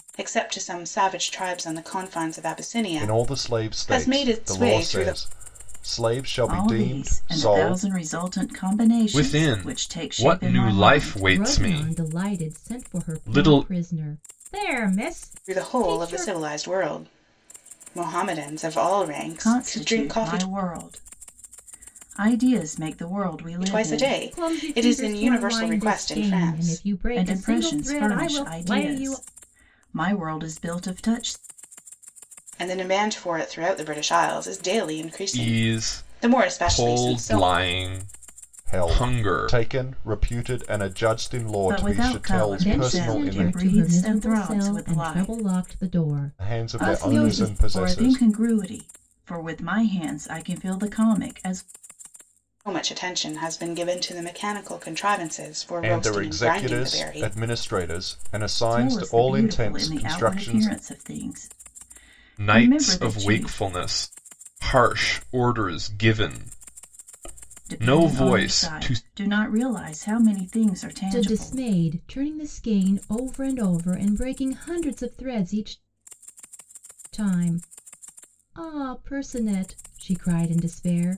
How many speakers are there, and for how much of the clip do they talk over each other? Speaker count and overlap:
5, about 38%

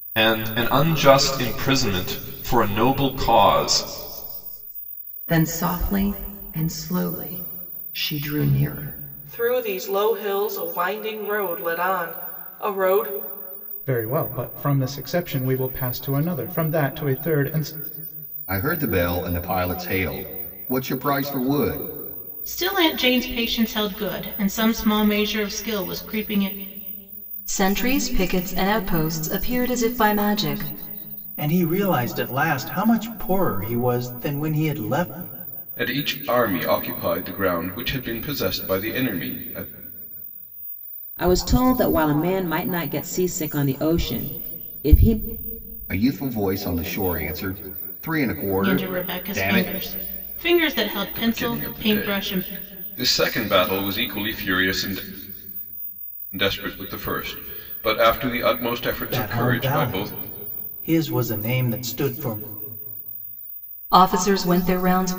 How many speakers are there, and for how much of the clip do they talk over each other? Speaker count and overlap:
10, about 6%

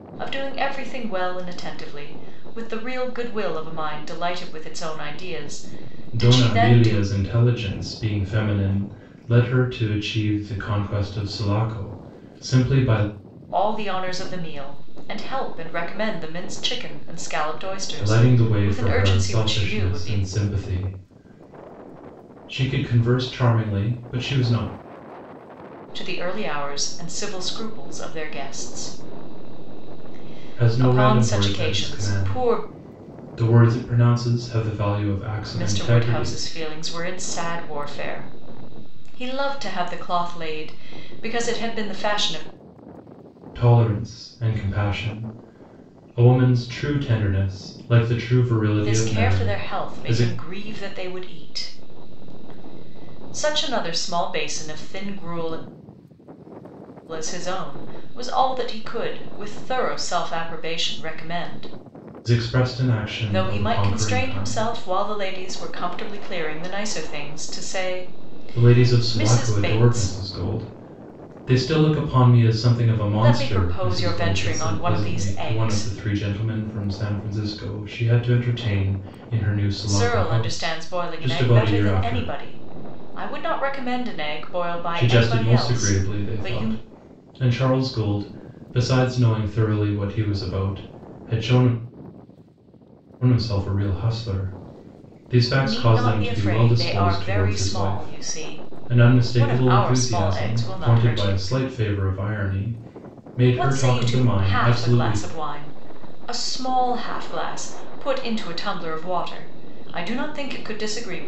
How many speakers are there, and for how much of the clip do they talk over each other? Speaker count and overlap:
2, about 22%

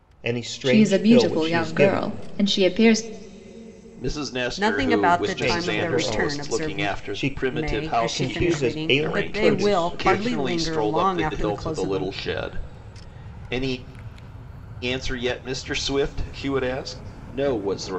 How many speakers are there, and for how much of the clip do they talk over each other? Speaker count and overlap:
4, about 50%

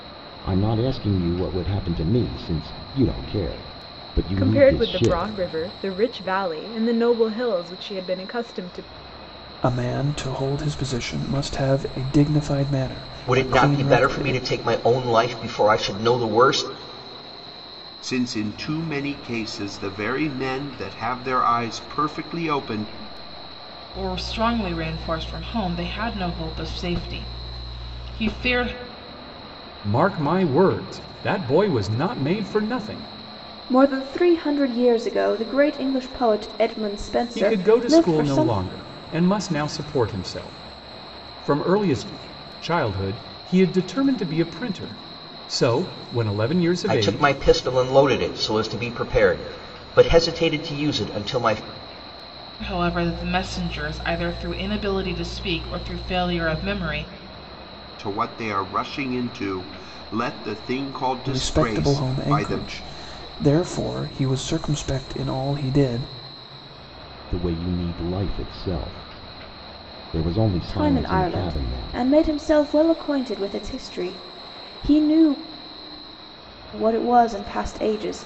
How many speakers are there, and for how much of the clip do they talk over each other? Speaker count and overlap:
8, about 9%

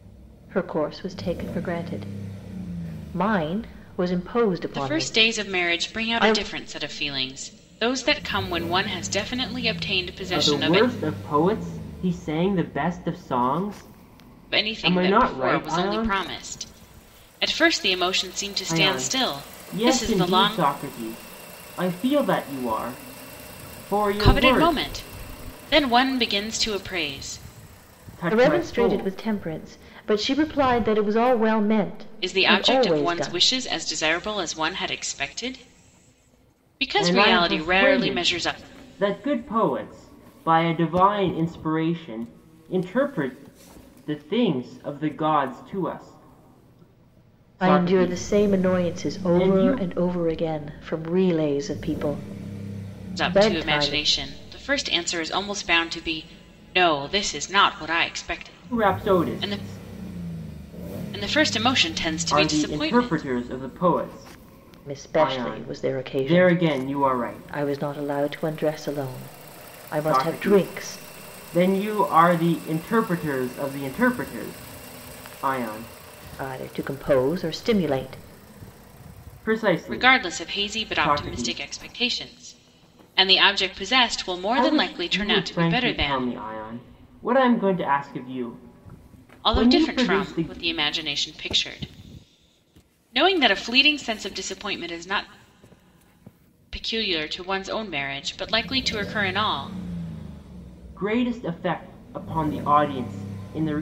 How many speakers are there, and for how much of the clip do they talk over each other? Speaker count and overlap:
3, about 23%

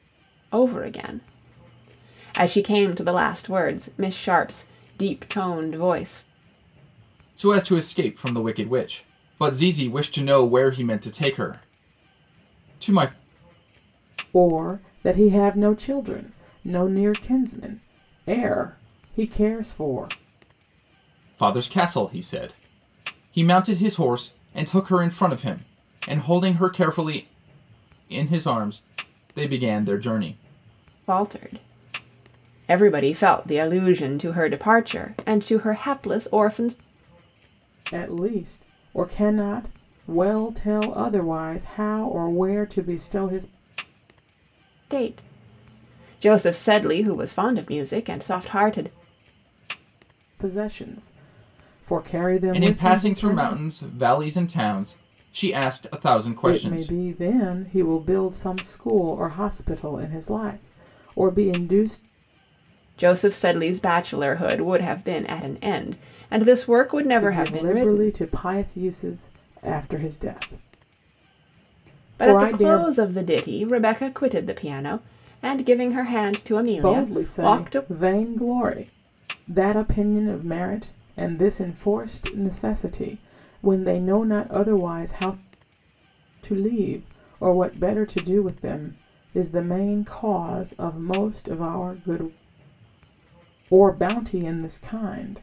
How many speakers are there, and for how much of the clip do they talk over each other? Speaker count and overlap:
3, about 5%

